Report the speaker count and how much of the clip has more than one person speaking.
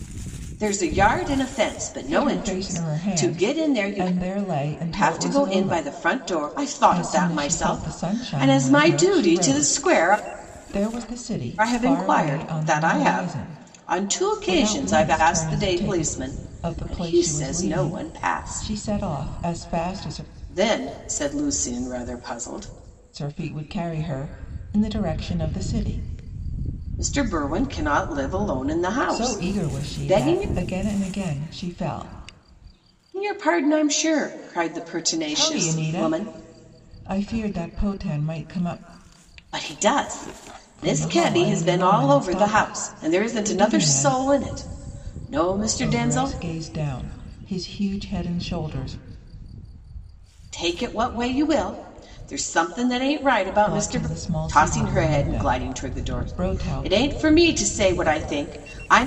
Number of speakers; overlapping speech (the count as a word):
two, about 40%